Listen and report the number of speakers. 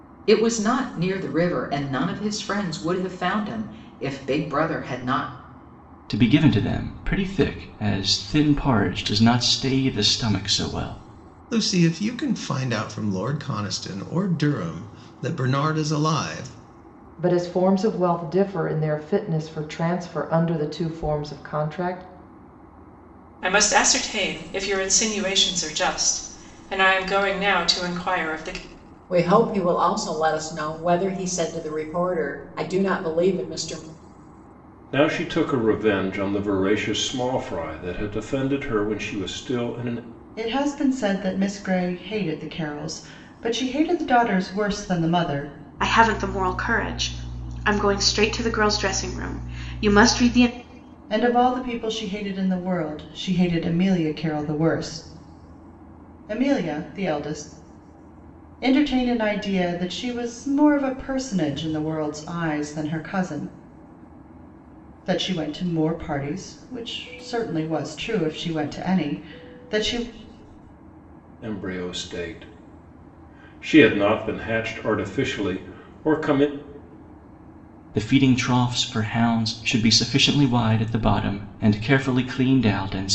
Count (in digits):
9